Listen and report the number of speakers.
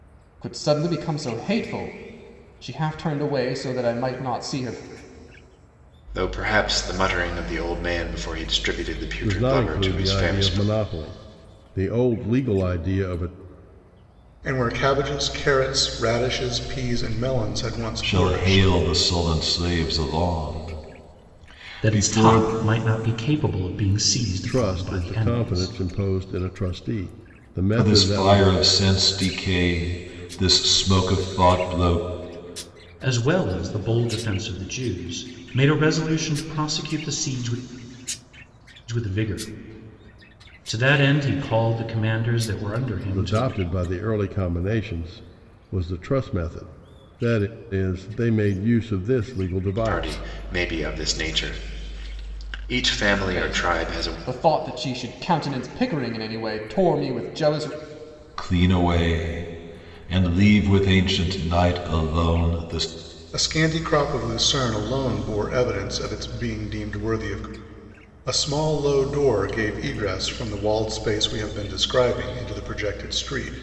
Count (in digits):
6